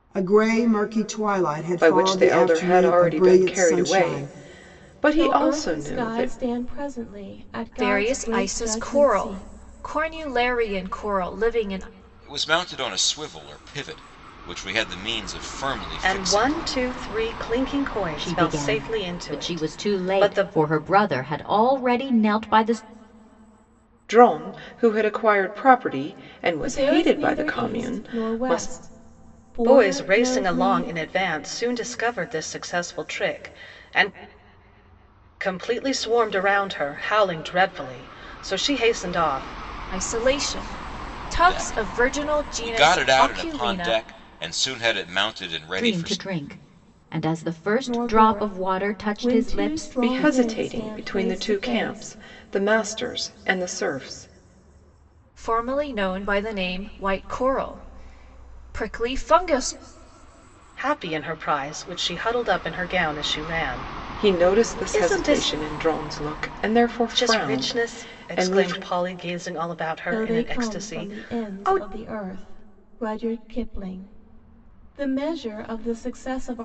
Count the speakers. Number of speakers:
7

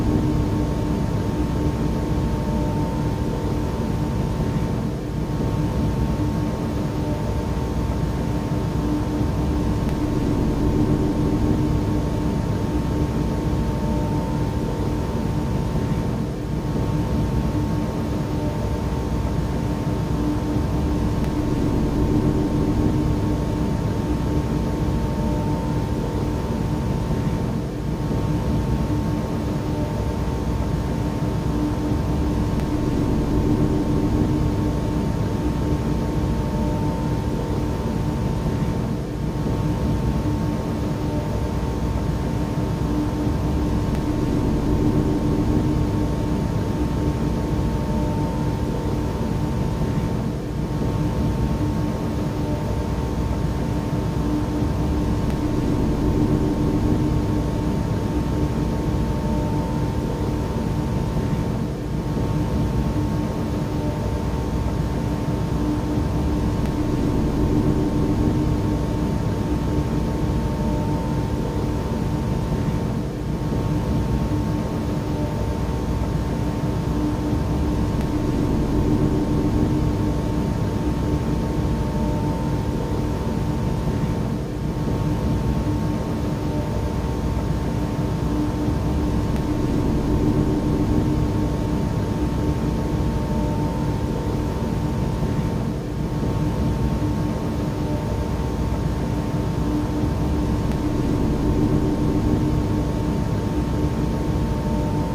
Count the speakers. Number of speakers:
0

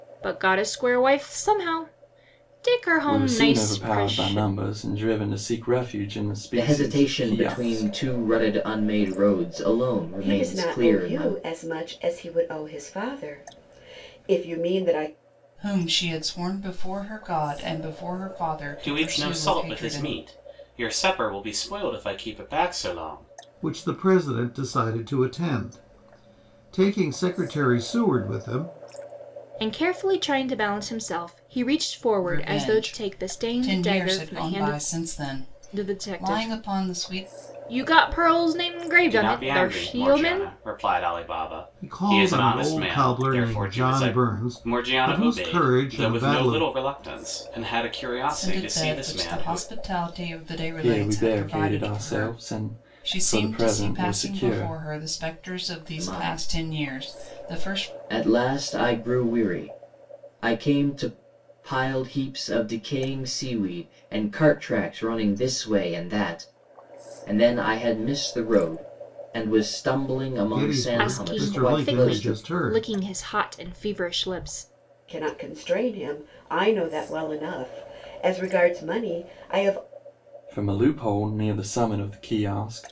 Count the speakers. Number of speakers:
7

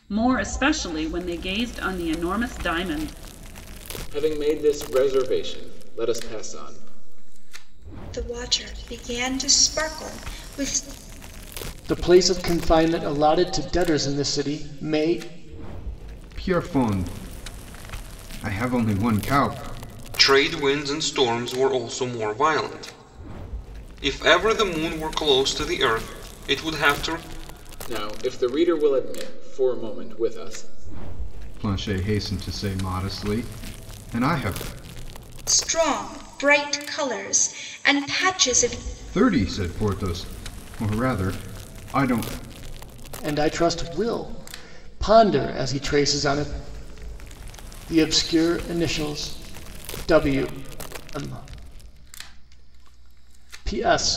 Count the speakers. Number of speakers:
6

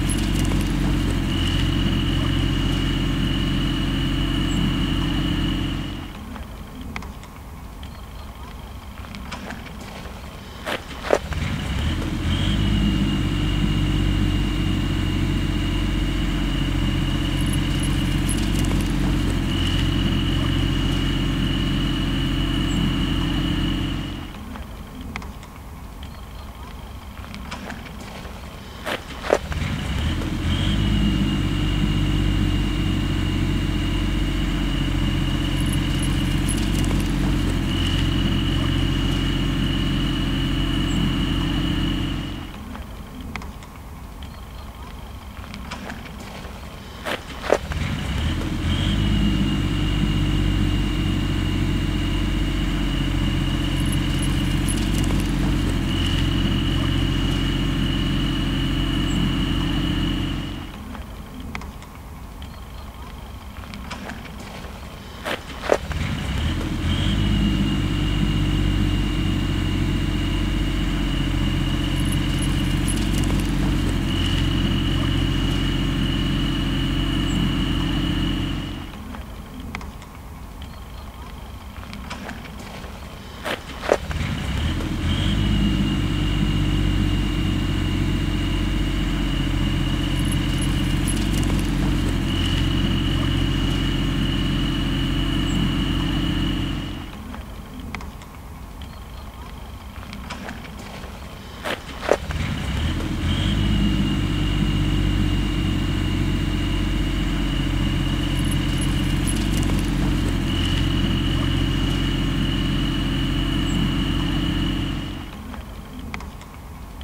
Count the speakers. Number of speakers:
0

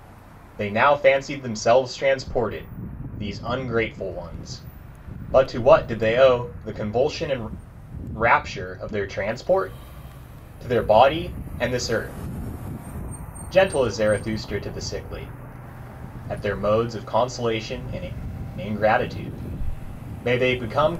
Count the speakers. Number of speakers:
1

